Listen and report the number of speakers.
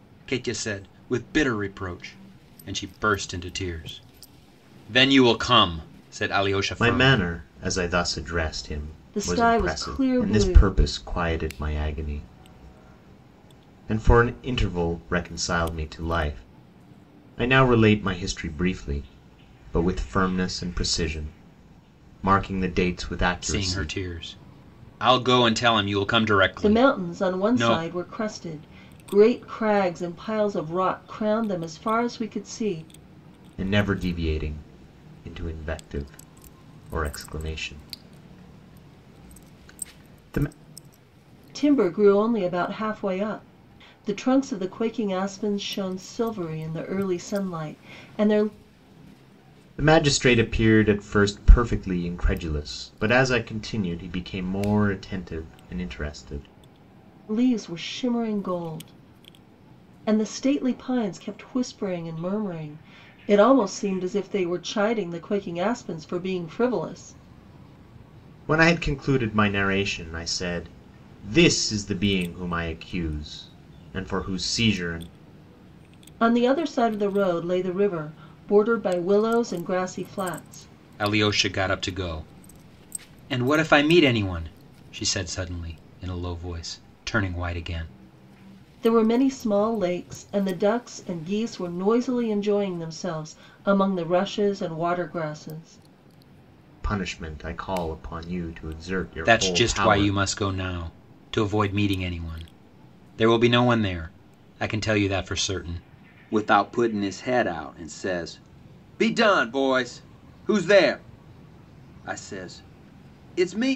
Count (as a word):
three